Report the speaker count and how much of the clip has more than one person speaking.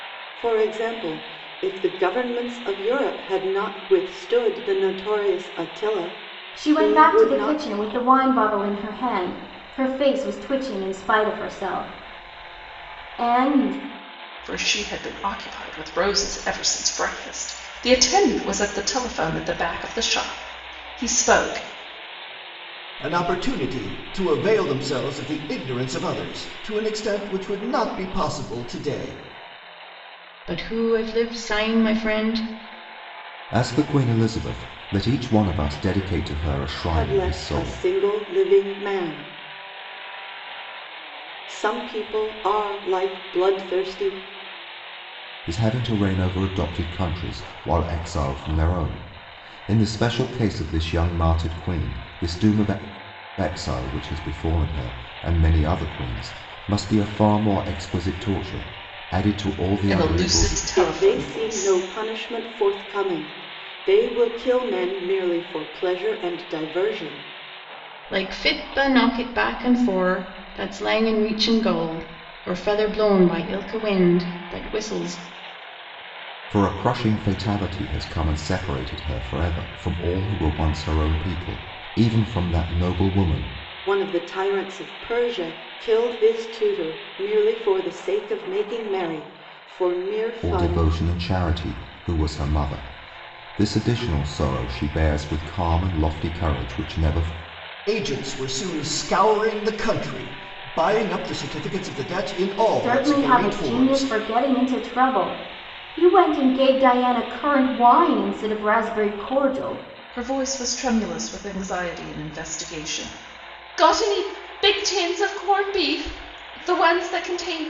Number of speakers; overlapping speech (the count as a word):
six, about 5%